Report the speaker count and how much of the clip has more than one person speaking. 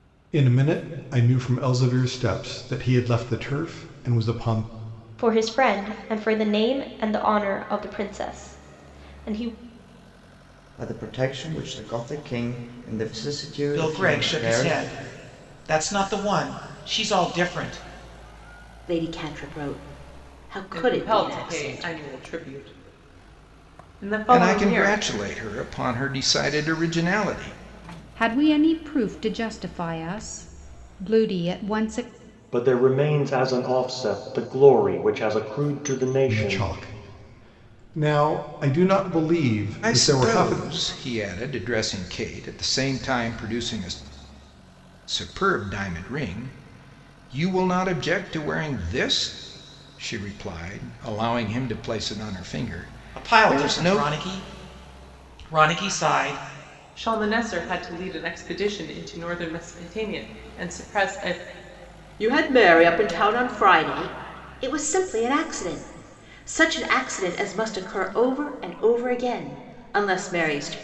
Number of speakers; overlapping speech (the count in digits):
9, about 7%